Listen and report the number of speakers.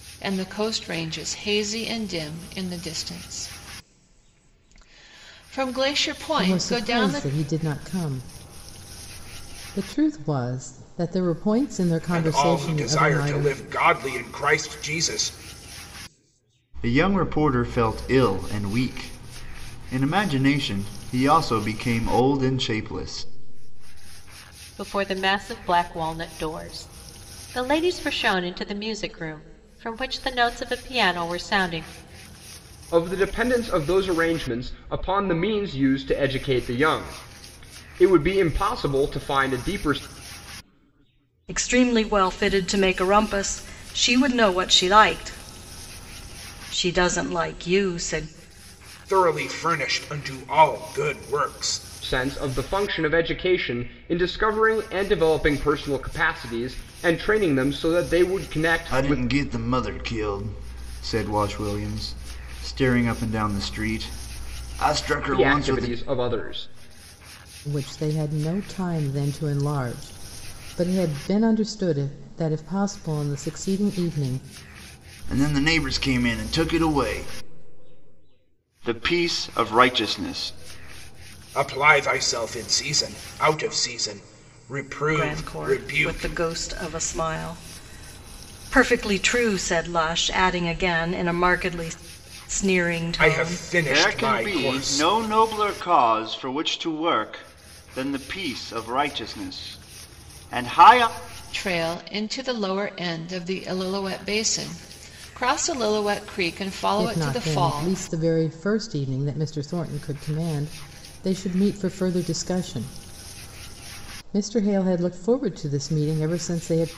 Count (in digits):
7